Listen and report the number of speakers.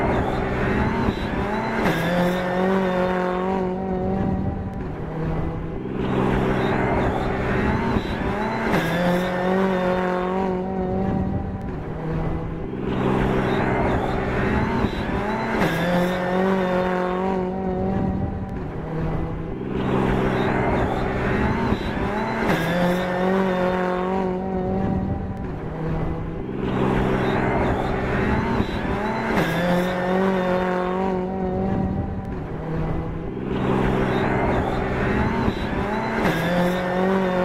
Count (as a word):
zero